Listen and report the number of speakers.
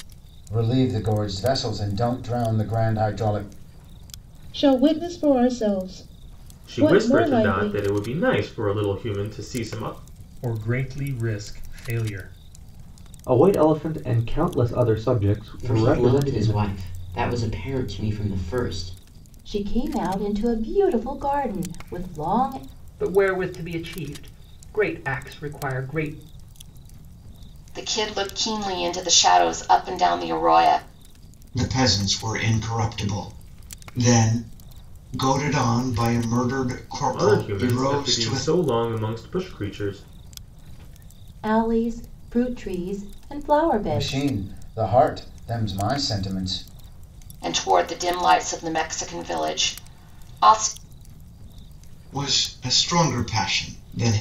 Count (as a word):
ten